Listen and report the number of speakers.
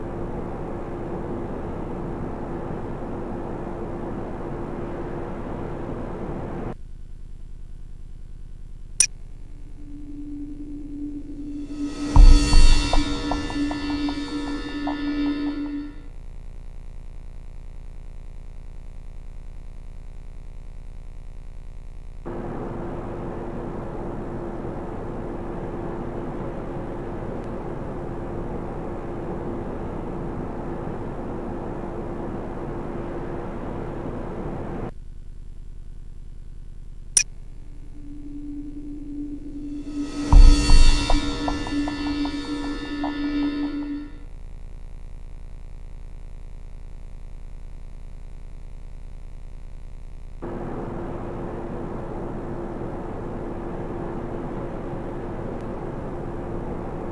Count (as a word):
zero